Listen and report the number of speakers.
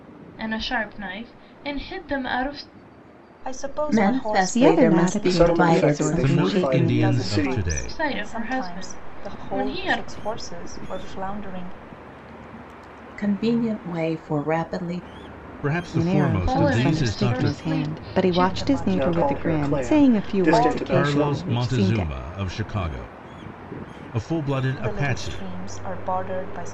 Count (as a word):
six